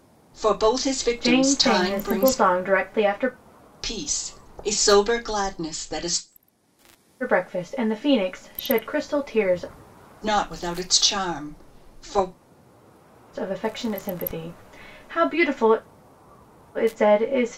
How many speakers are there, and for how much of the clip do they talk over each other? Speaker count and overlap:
2, about 7%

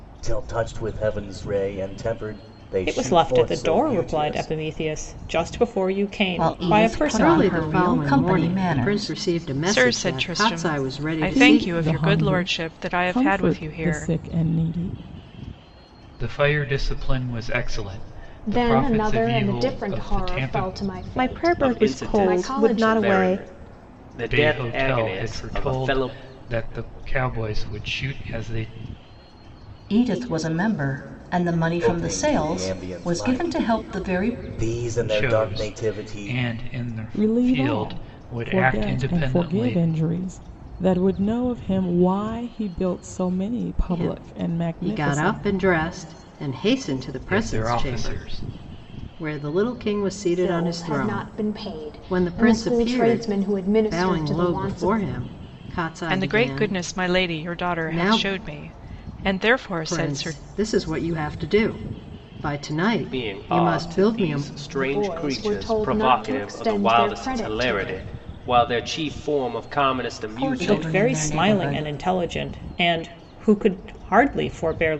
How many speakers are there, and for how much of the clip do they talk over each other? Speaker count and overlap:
10, about 50%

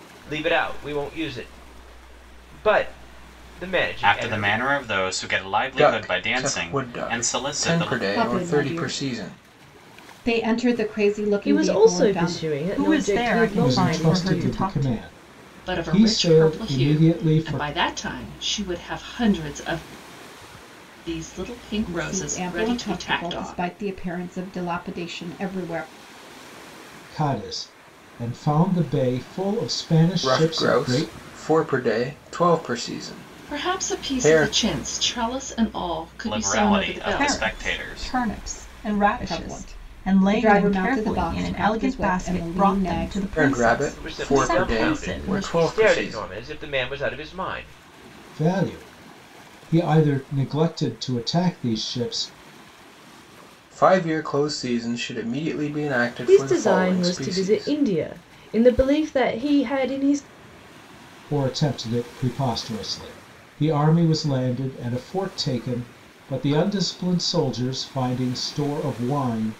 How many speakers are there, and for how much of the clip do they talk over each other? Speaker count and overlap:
8, about 35%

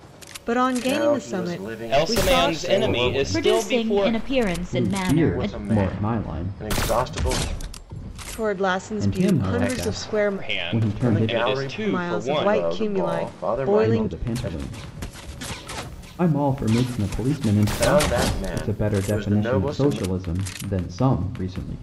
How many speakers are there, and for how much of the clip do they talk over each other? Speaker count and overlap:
5, about 63%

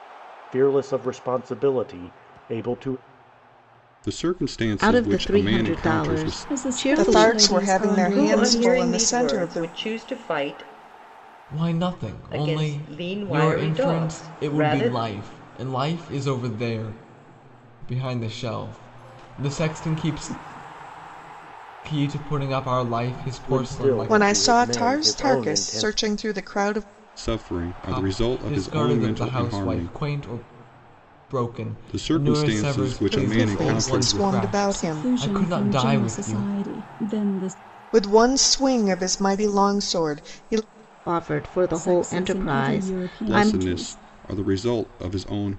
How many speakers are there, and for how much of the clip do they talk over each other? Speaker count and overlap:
7, about 42%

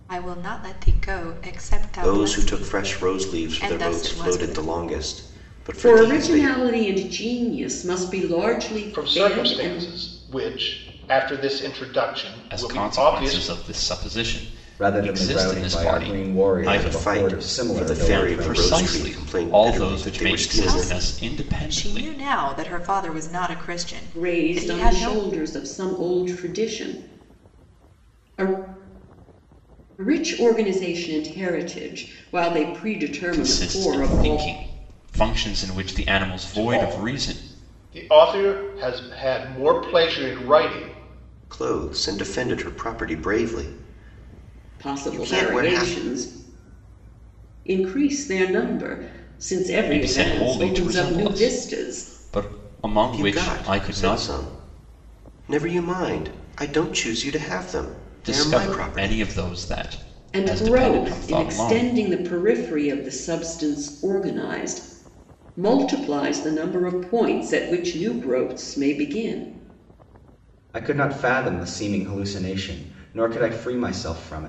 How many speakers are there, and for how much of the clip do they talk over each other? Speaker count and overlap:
6, about 31%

